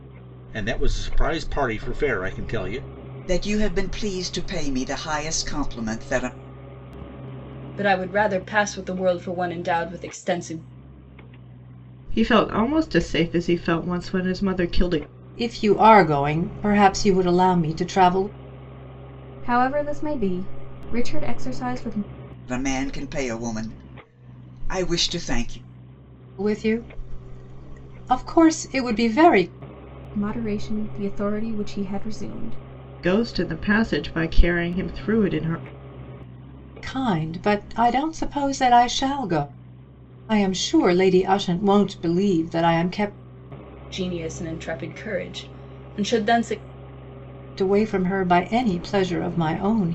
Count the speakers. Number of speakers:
6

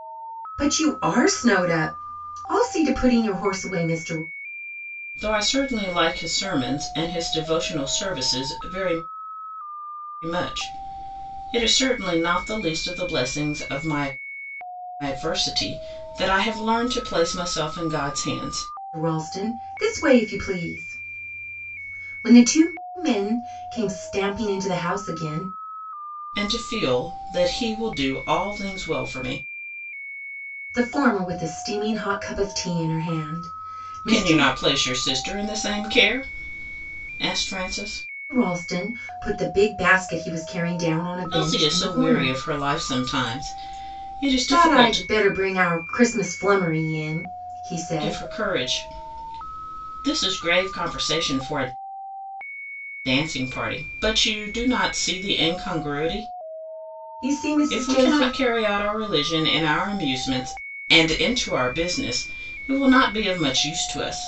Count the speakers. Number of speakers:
2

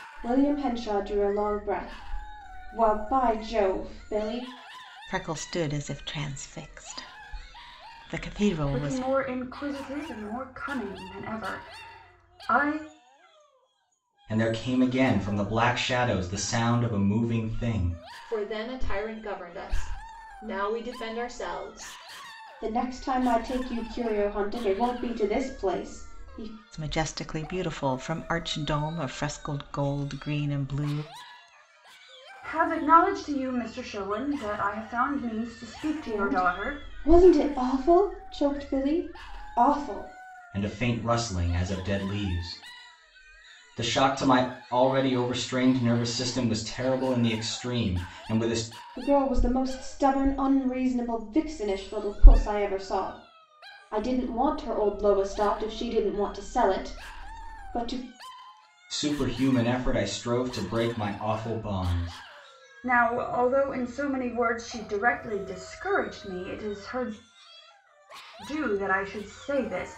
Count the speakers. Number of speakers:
5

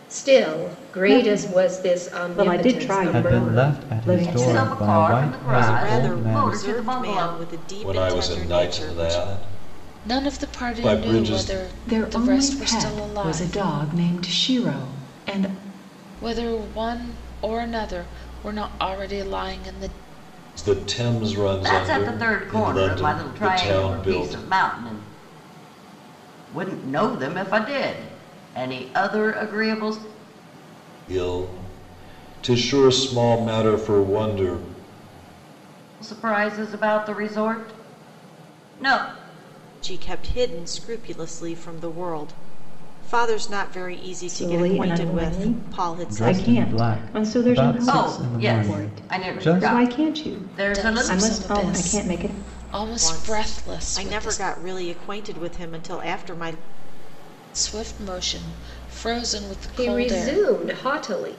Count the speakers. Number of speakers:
8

